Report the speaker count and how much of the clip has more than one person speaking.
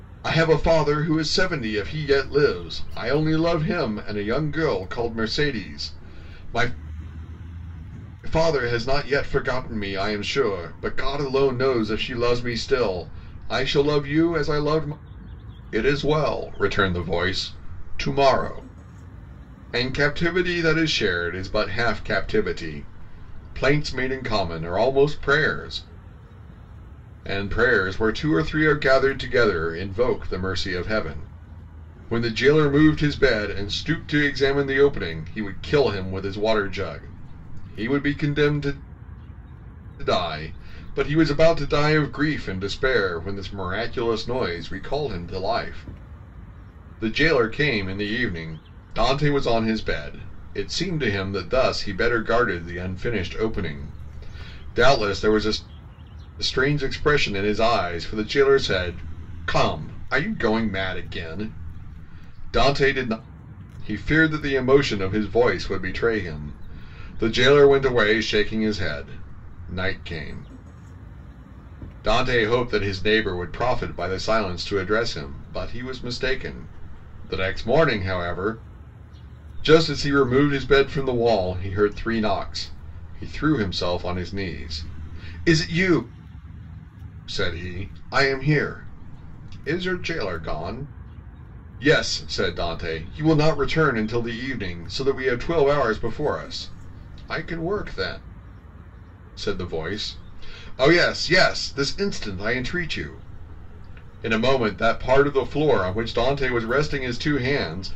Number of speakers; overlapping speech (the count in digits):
1, no overlap